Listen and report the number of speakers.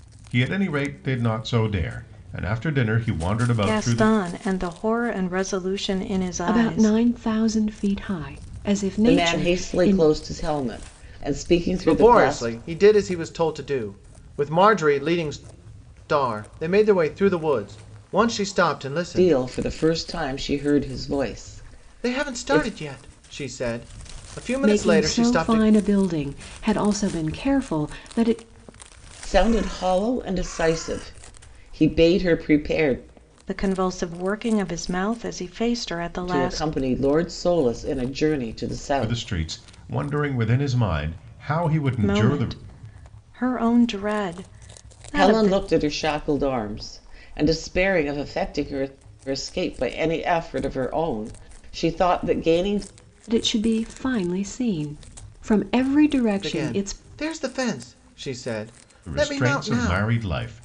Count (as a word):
five